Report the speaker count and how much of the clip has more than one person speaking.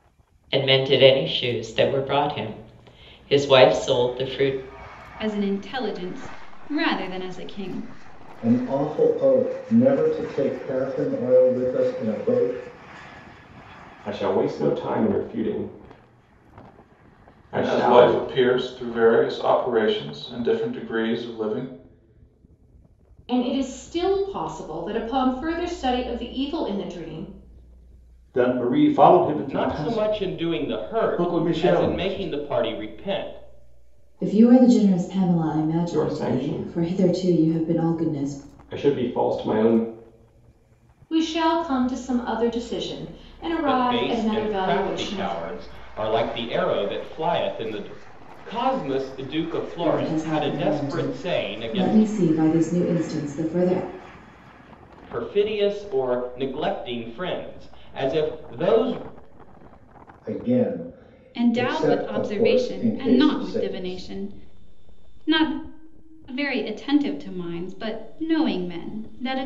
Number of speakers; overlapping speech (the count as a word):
nine, about 19%